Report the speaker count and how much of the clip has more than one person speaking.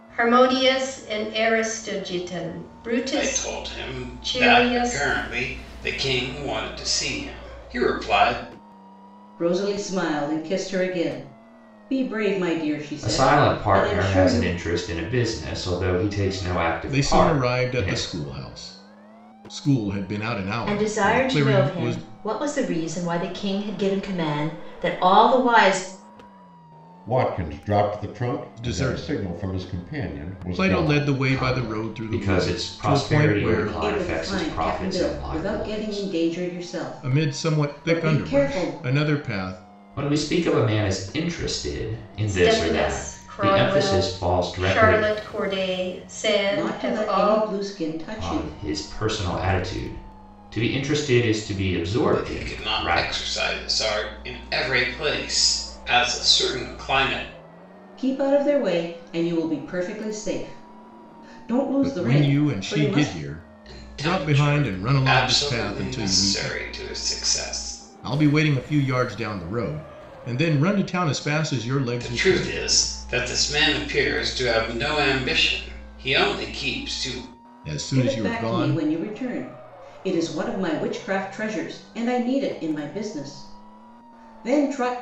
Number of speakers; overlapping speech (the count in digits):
7, about 32%